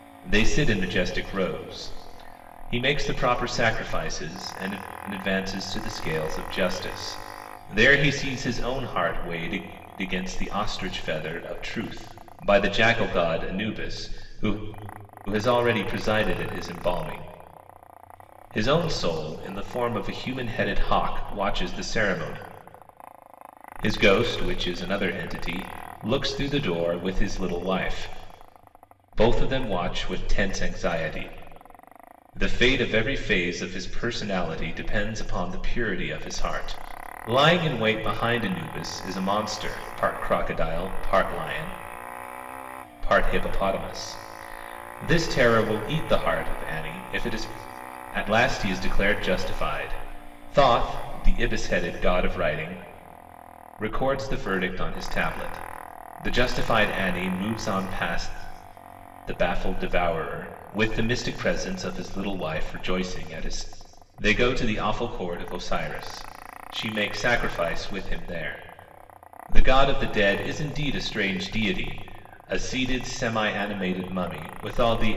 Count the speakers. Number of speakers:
one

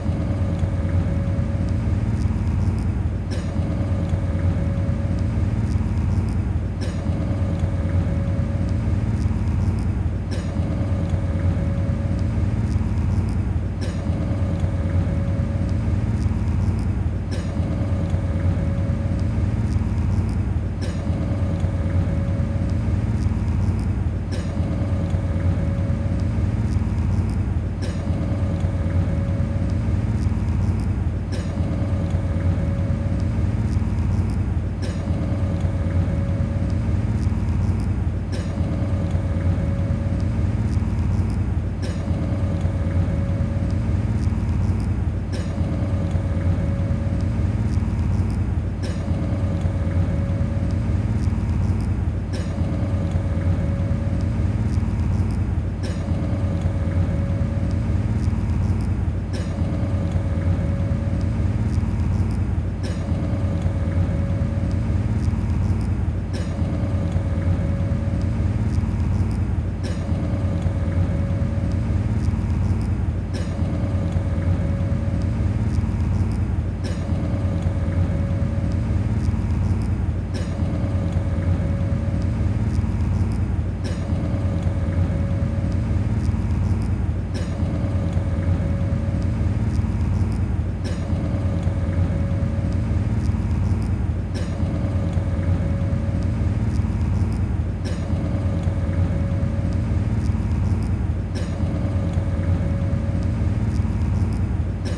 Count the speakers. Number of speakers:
zero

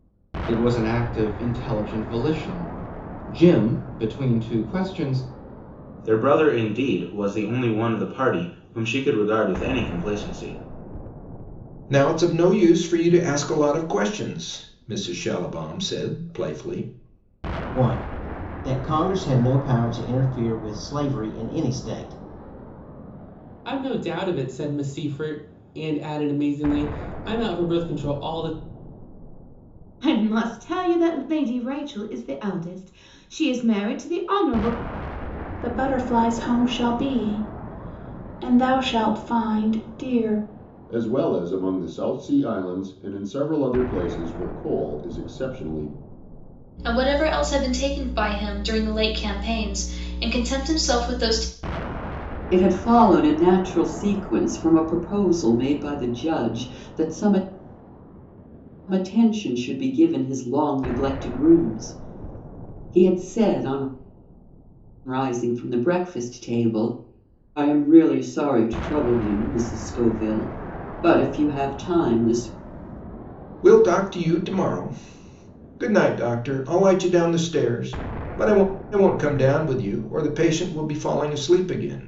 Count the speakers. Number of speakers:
ten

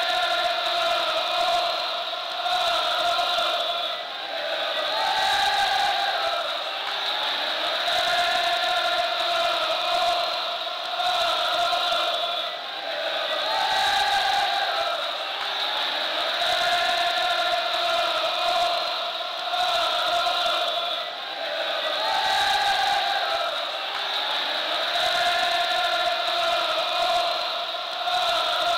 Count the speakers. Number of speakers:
zero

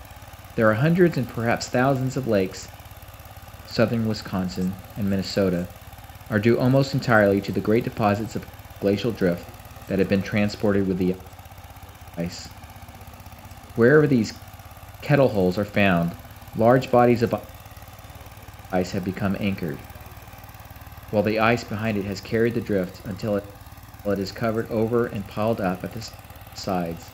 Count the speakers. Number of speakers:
one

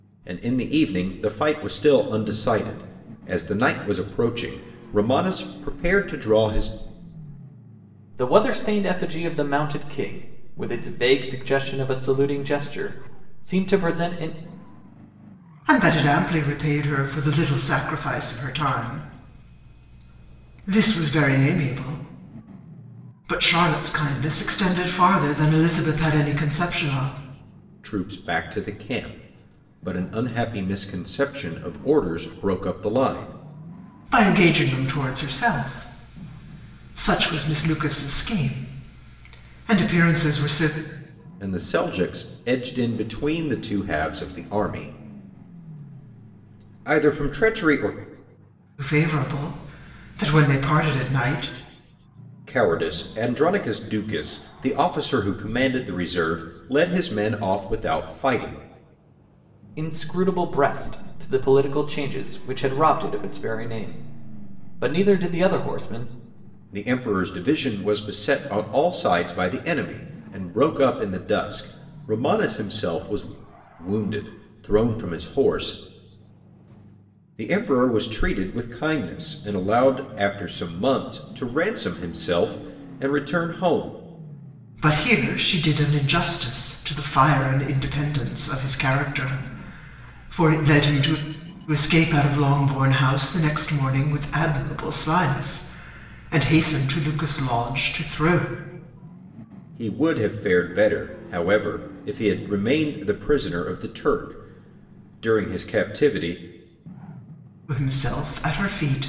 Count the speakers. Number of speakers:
three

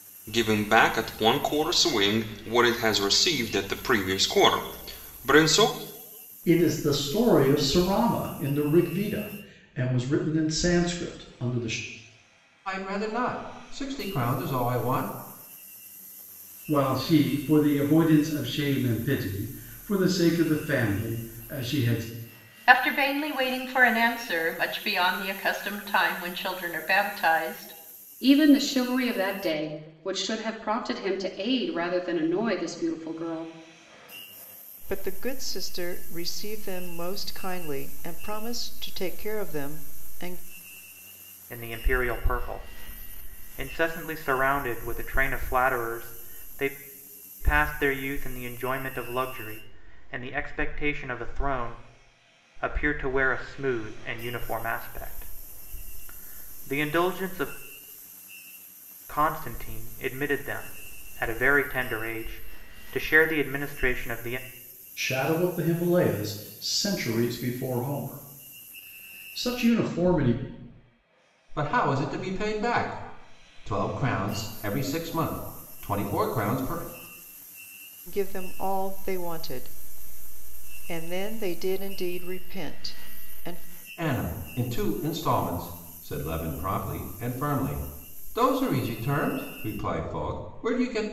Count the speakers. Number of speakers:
eight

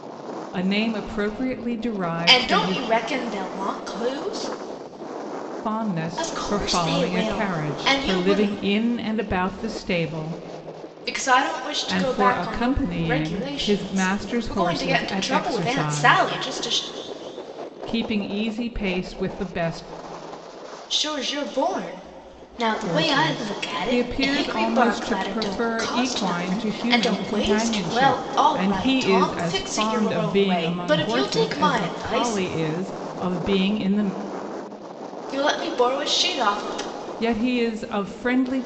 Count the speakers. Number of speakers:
two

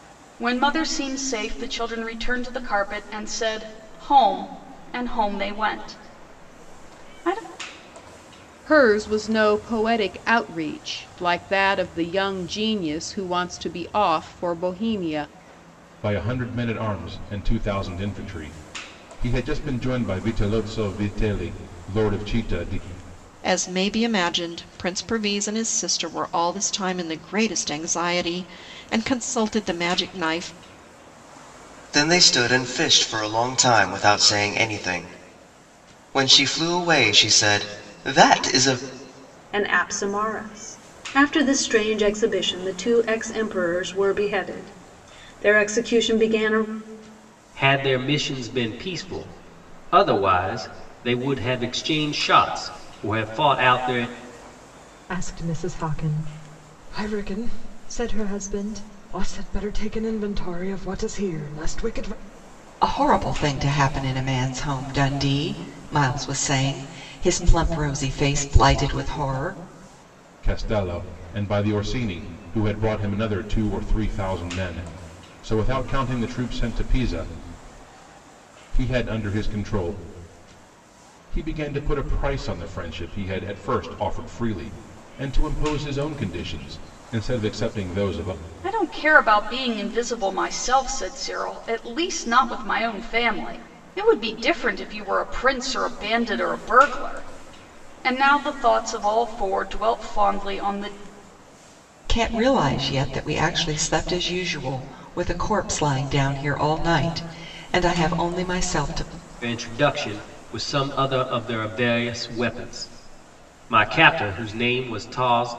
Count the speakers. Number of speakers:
nine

